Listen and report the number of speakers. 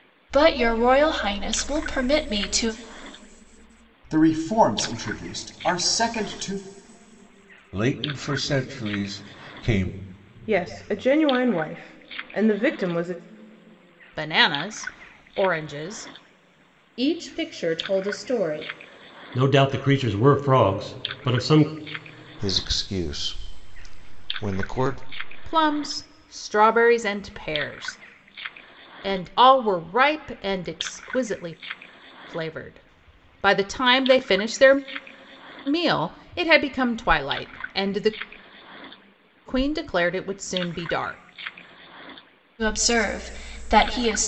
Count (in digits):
8